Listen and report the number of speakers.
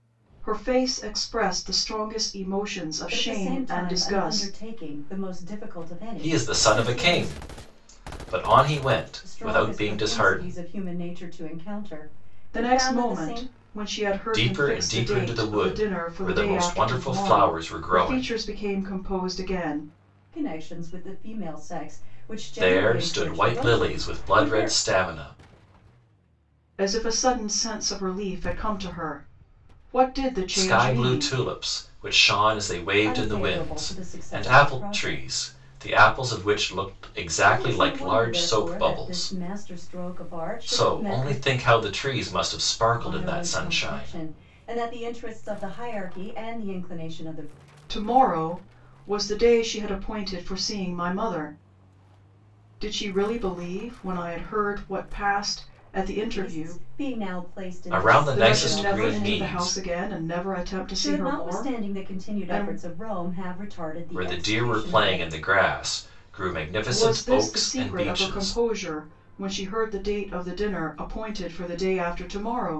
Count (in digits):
3